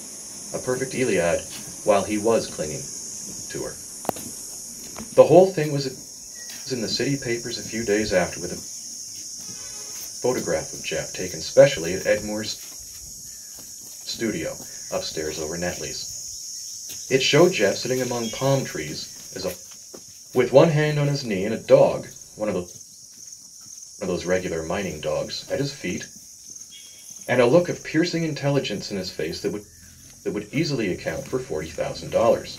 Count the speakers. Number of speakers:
one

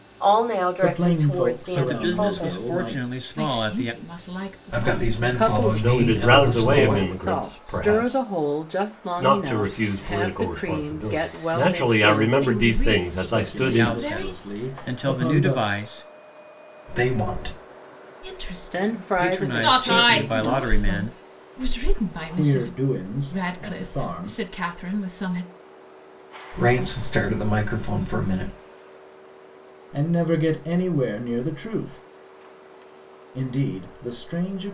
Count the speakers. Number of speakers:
seven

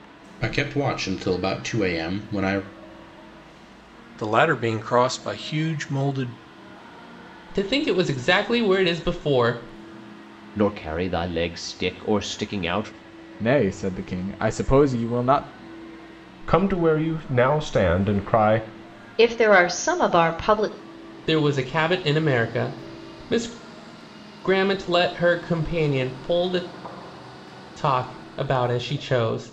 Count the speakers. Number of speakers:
seven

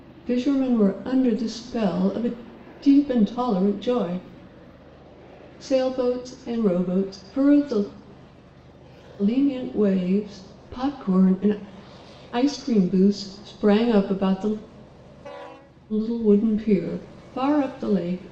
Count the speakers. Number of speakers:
one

